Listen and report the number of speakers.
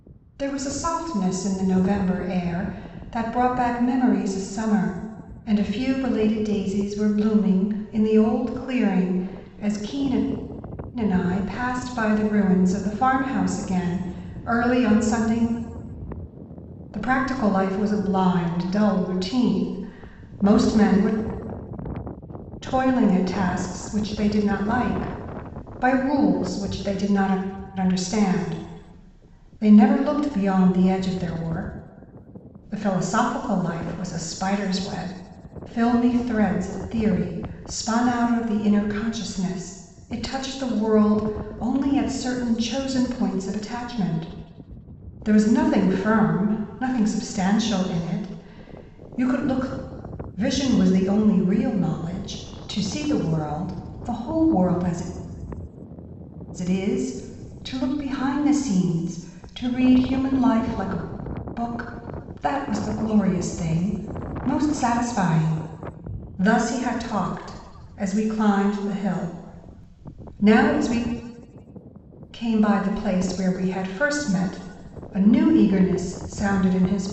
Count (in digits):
1